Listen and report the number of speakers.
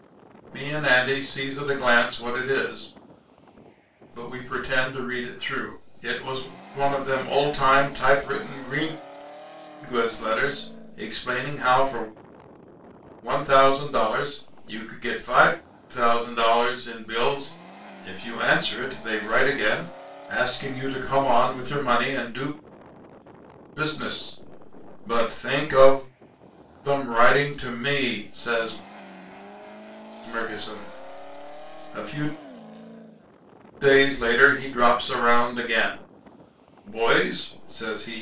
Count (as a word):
one